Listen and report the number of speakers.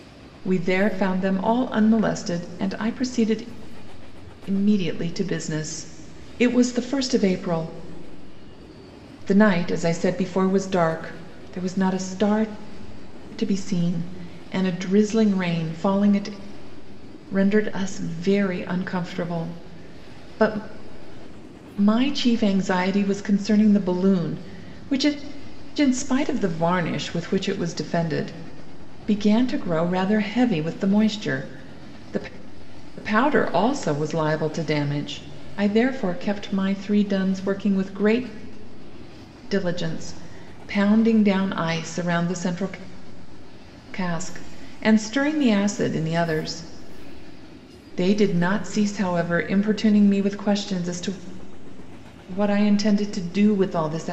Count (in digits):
1